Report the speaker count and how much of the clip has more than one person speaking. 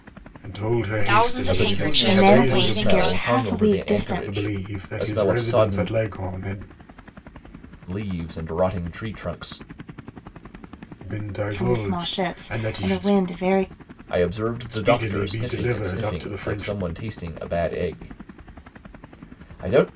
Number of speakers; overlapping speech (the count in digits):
4, about 44%